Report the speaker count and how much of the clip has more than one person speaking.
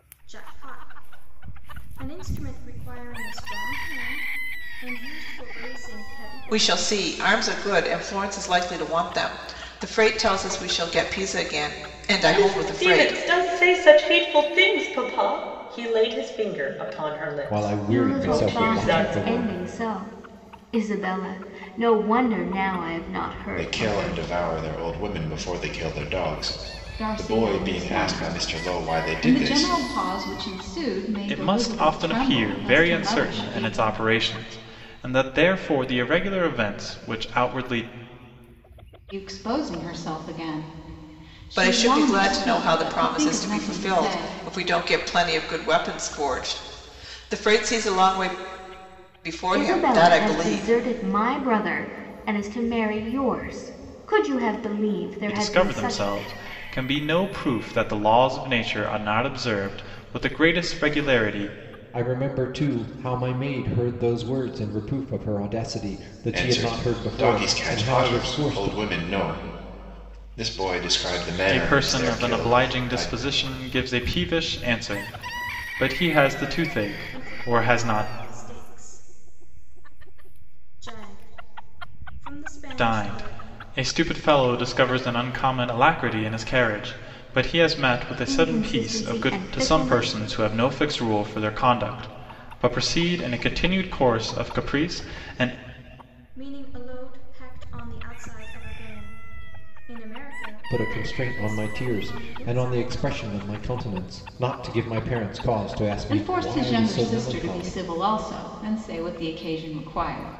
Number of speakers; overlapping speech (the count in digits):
8, about 24%